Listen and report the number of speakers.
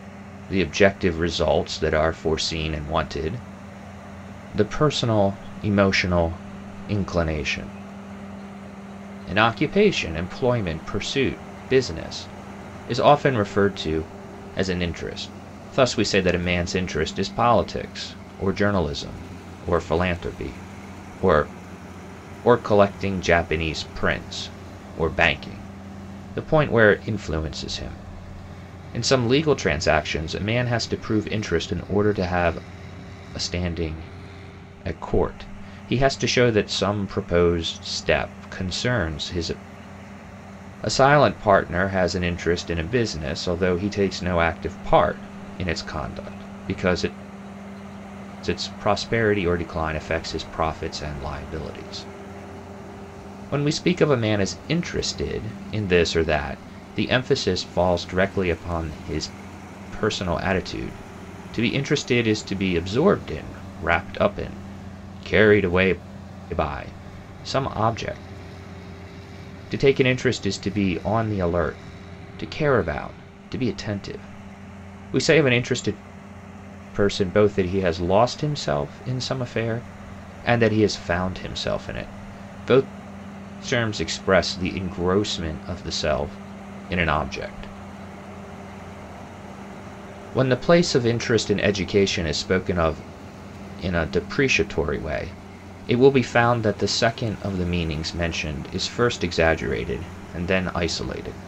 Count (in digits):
1